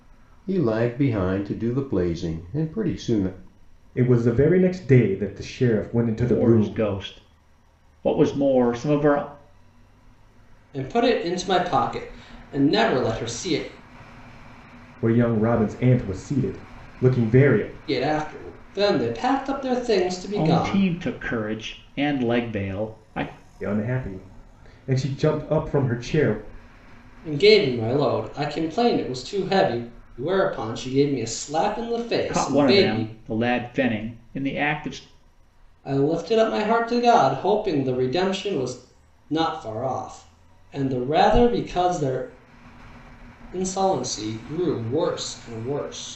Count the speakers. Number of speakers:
four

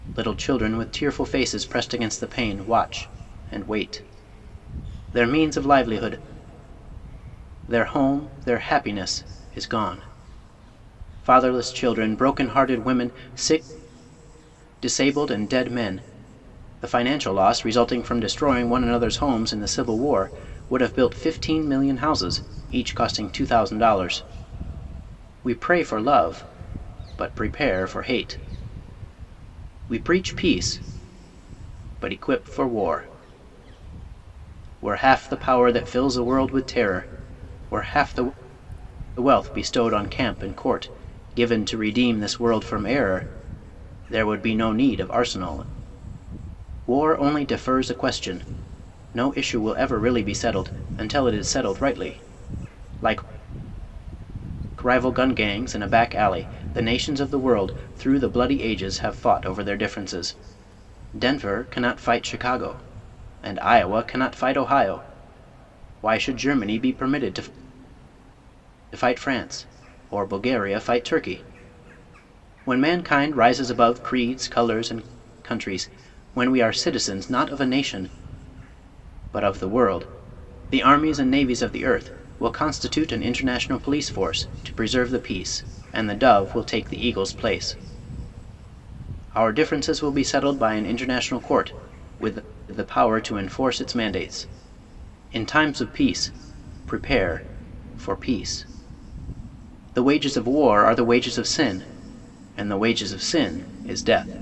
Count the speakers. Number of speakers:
one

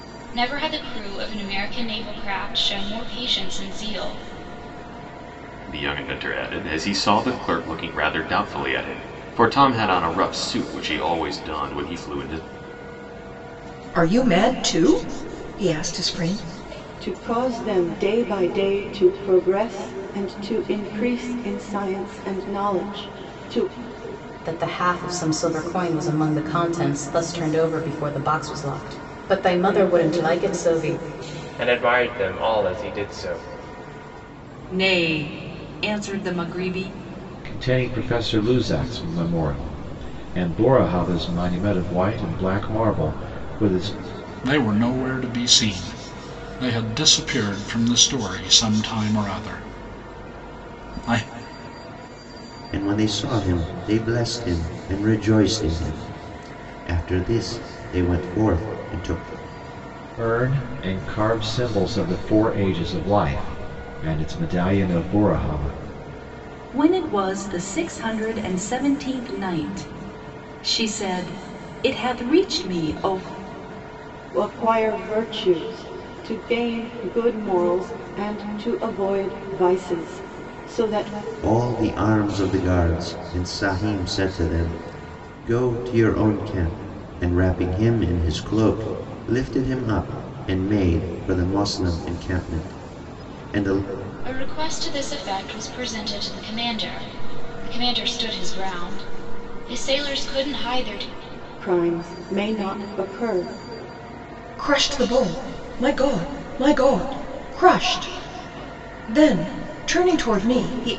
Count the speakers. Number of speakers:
ten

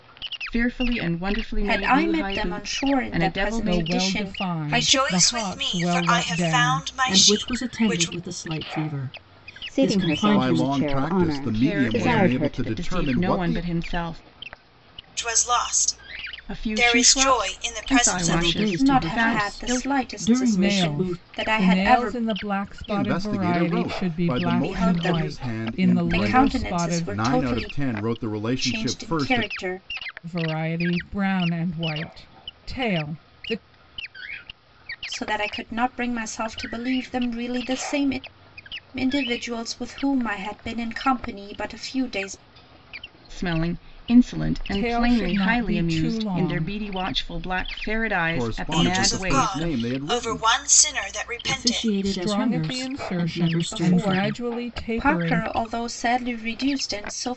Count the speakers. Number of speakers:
seven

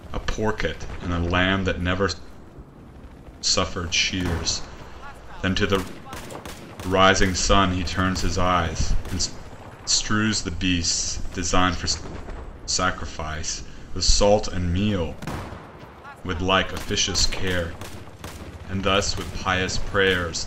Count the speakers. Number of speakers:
one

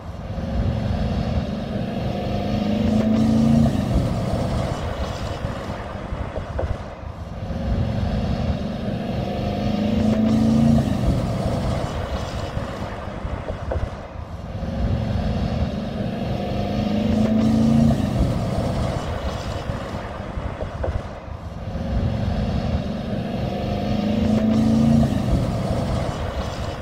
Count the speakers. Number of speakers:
zero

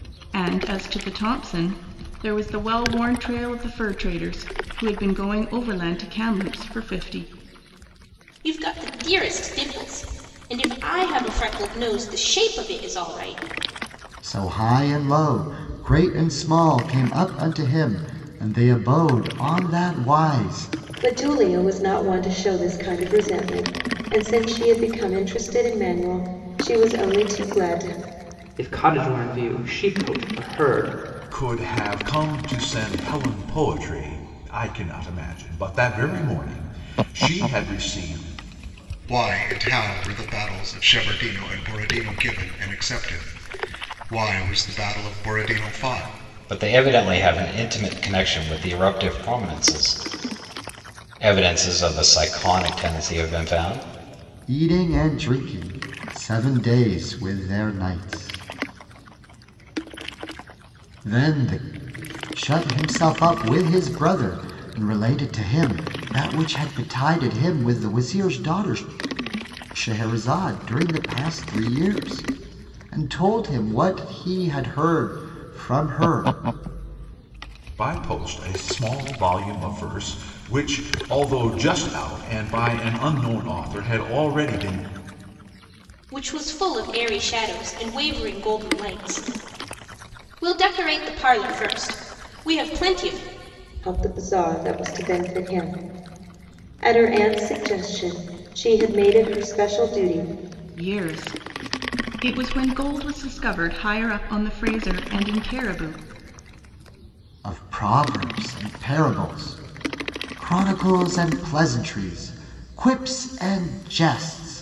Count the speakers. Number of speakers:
eight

